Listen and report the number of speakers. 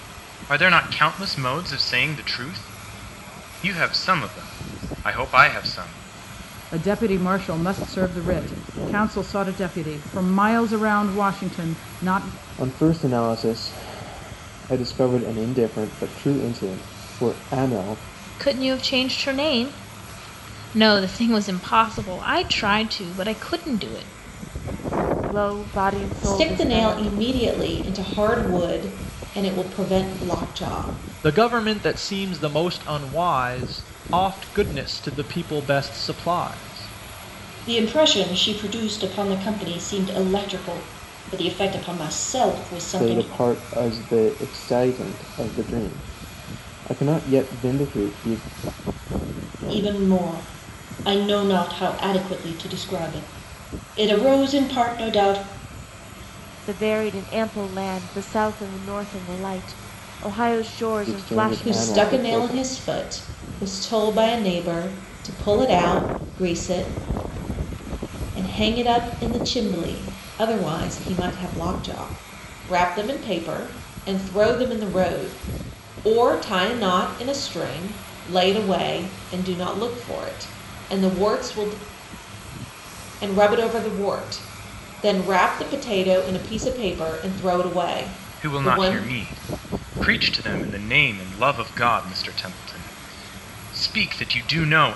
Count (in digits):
8